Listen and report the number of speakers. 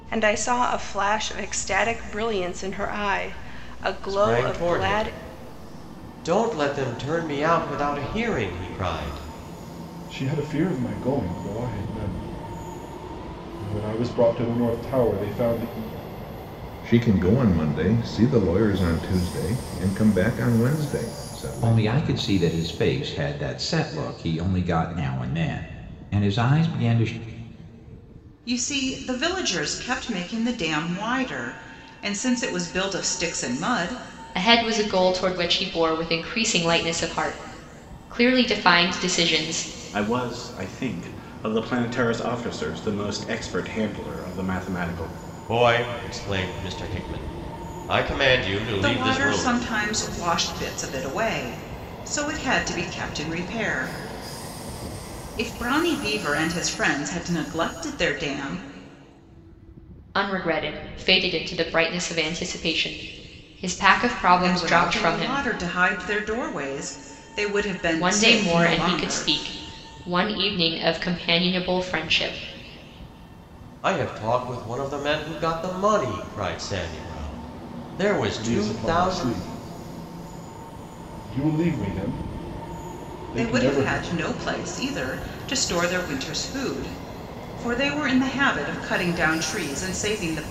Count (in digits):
8